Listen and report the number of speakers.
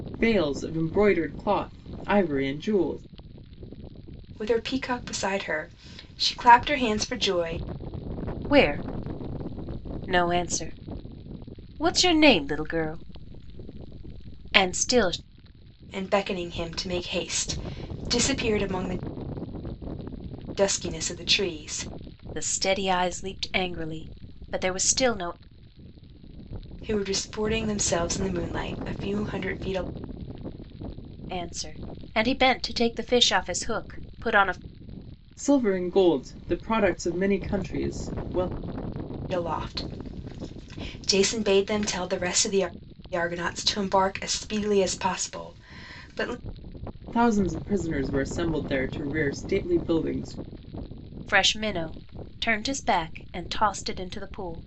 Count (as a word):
three